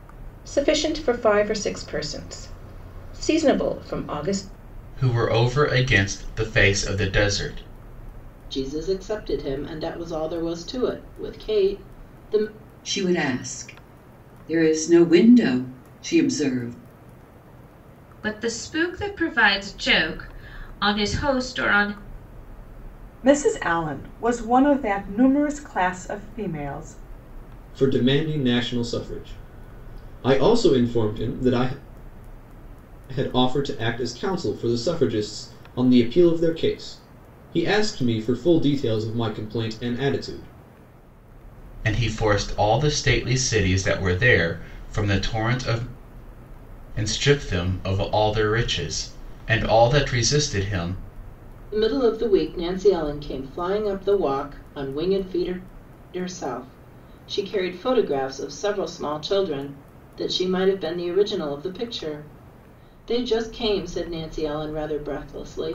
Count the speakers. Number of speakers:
7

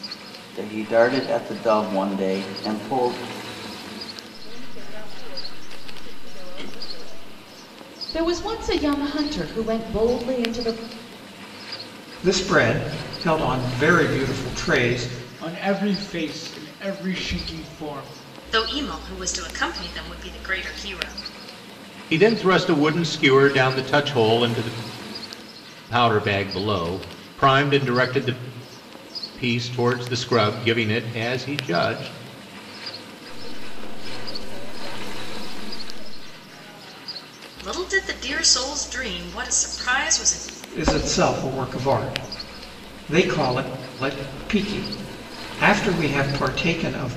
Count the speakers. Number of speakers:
7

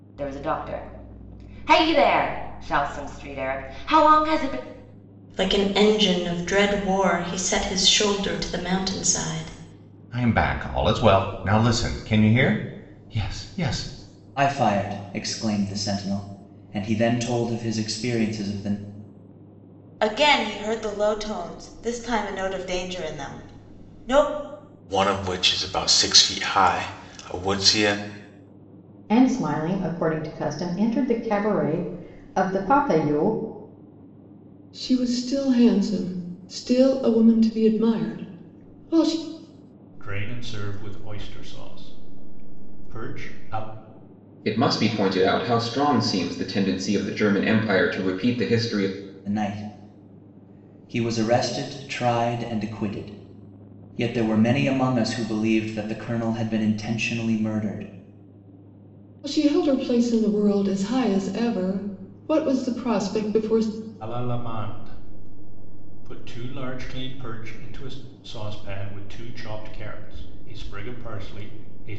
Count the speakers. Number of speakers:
10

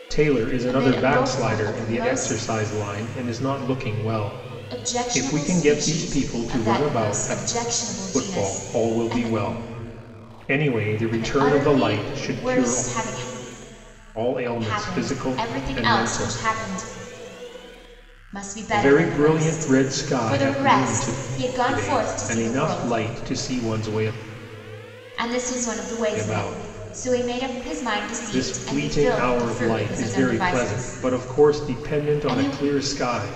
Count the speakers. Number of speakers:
2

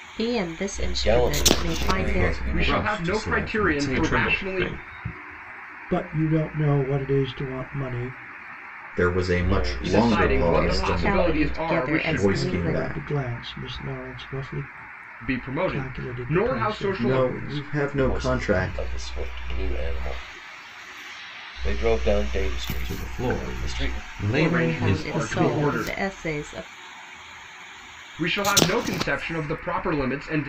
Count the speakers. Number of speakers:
7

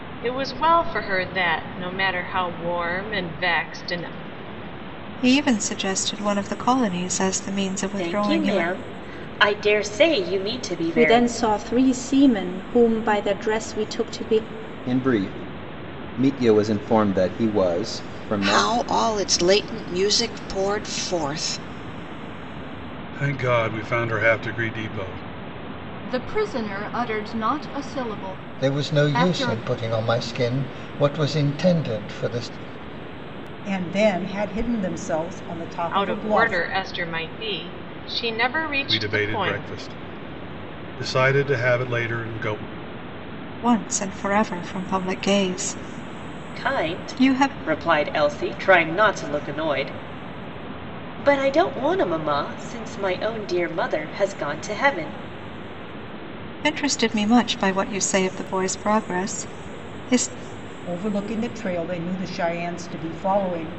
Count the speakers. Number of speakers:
10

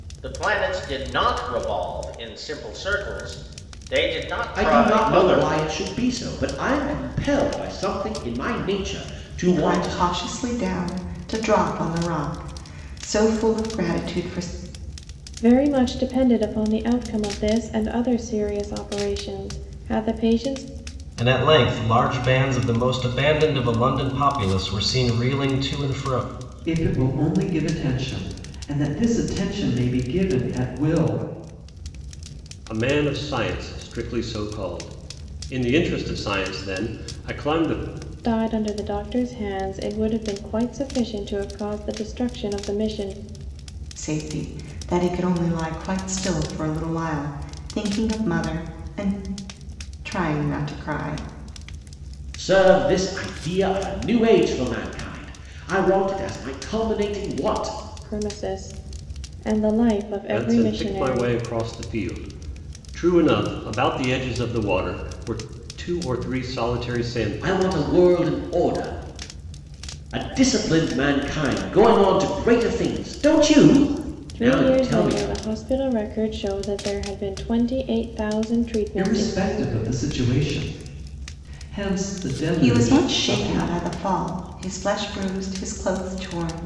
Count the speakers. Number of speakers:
7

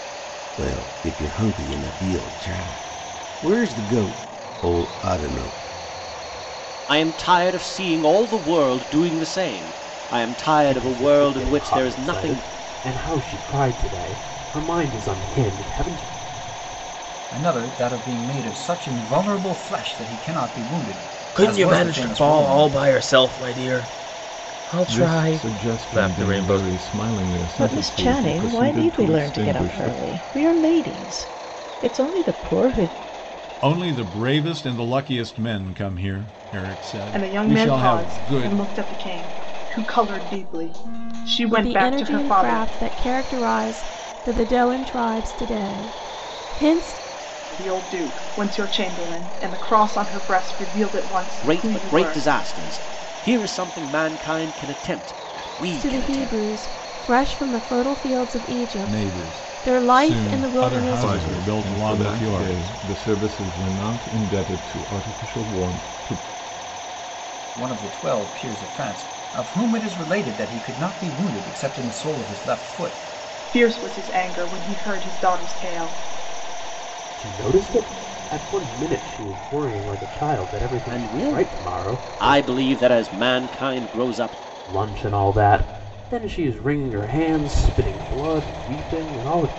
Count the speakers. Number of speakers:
10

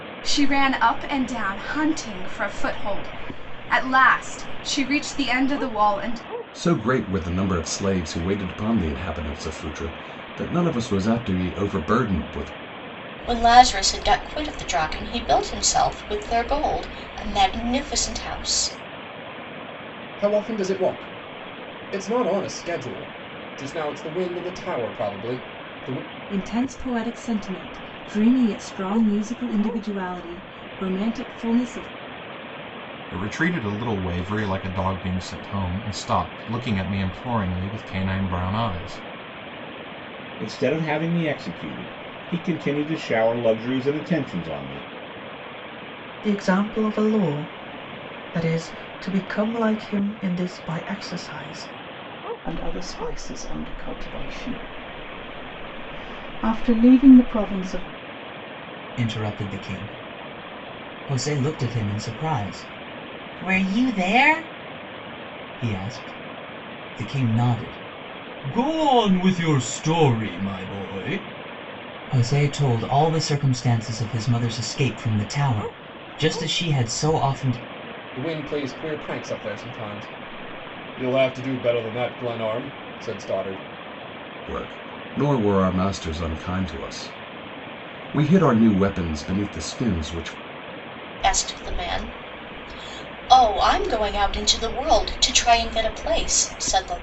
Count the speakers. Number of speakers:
10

